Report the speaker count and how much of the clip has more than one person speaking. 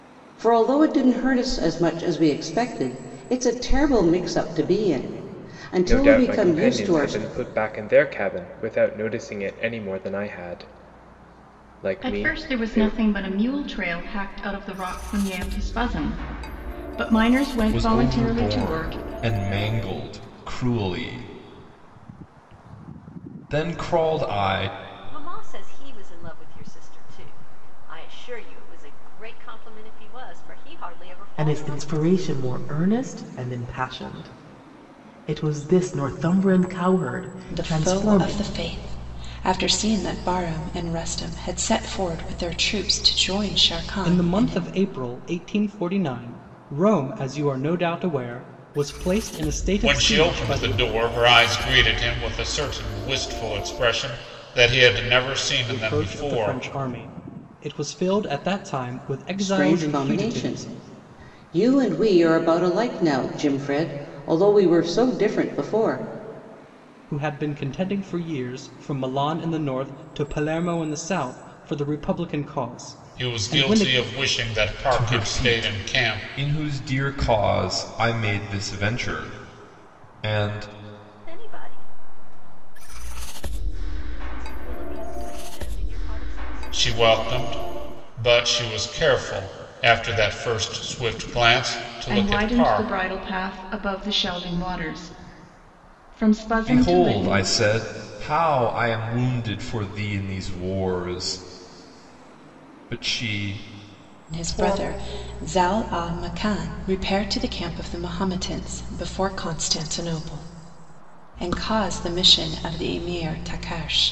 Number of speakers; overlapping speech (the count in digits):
9, about 12%